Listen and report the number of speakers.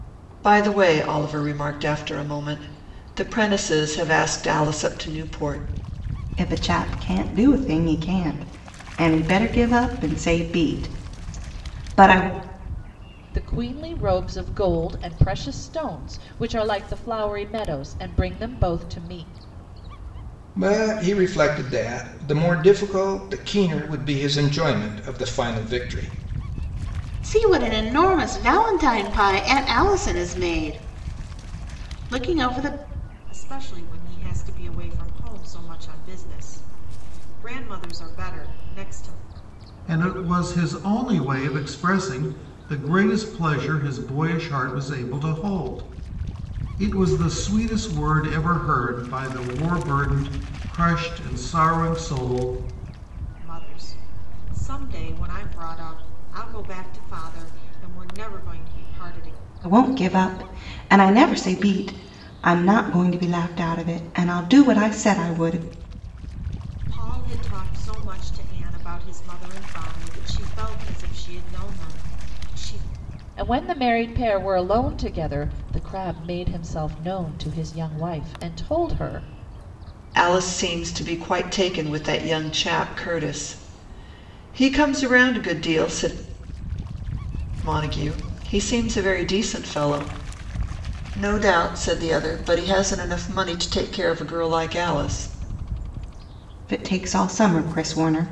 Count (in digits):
7